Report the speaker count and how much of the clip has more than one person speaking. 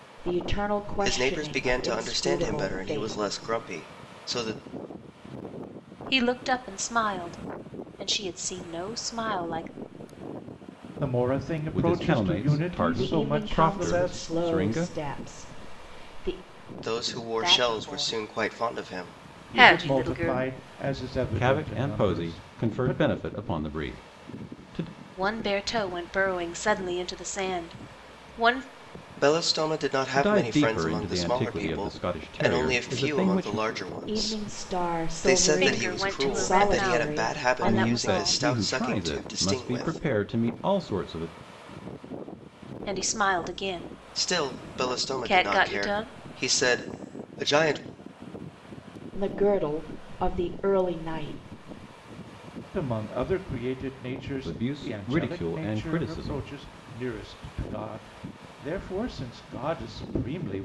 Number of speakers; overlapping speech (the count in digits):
5, about 39%